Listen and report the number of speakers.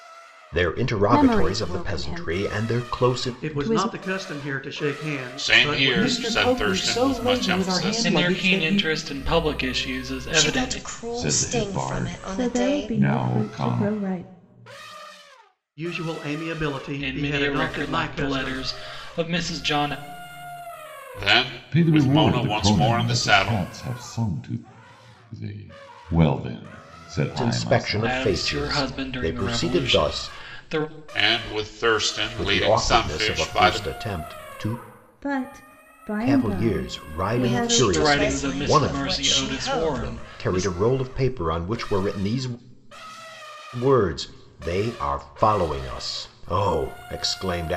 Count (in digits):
9